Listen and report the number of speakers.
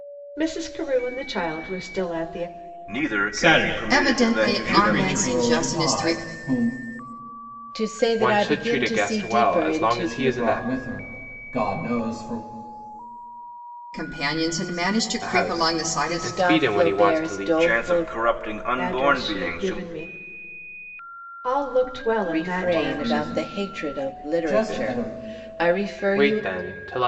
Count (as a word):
seven